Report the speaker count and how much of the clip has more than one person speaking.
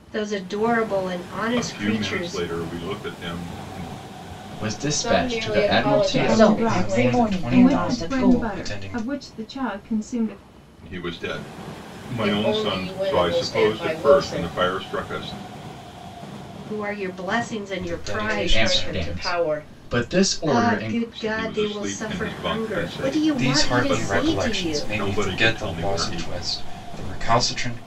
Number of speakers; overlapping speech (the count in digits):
7, about 53%